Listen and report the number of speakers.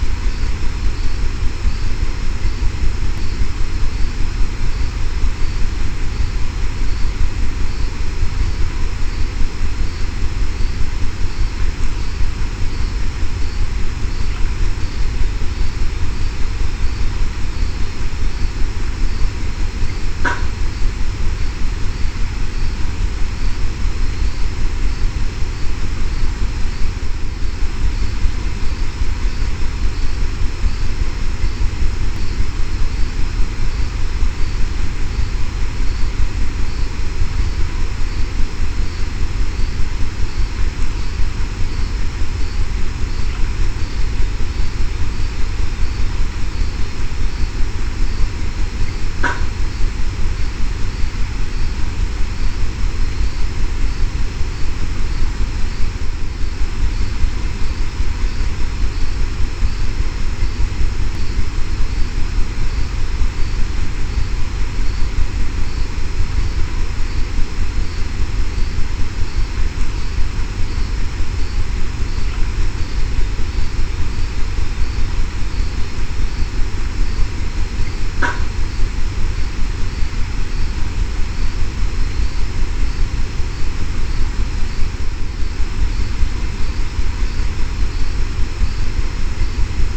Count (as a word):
zero